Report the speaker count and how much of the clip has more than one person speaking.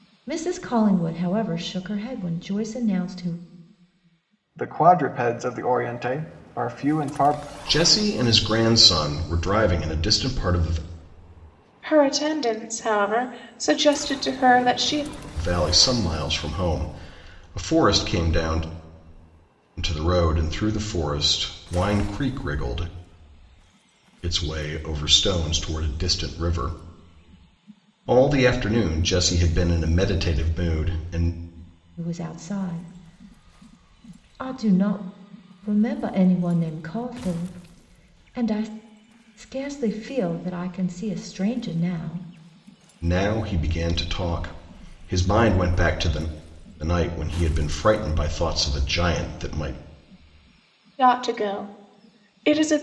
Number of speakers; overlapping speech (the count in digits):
4, no overlap